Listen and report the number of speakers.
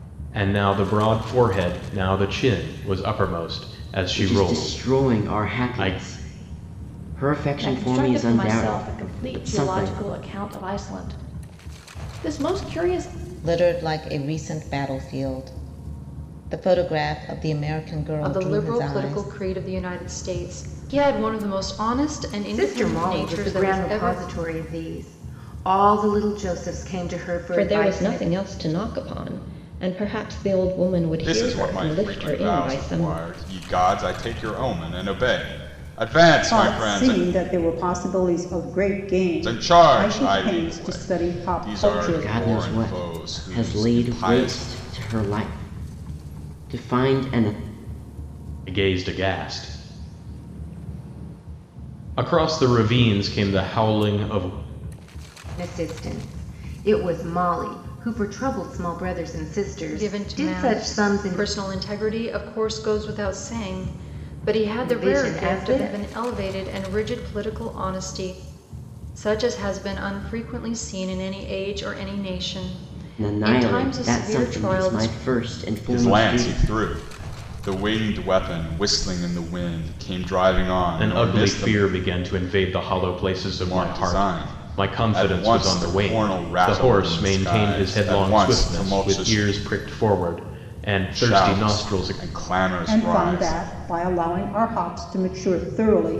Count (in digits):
9